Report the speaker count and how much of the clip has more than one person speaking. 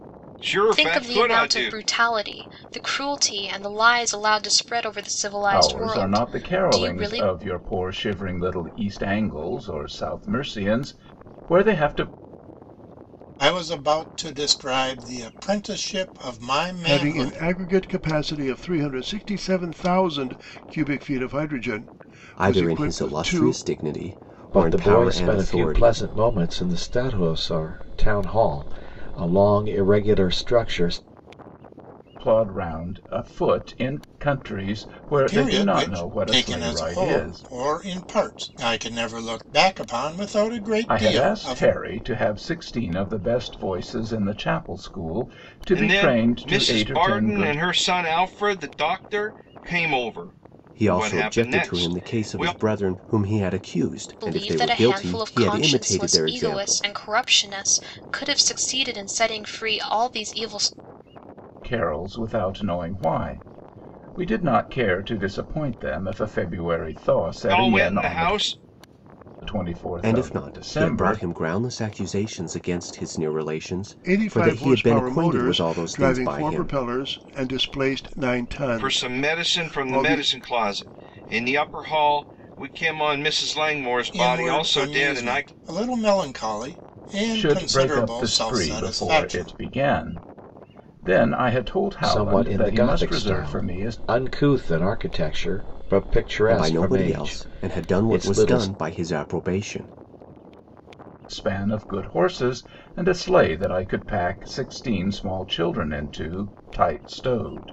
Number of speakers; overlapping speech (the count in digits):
7, about 28%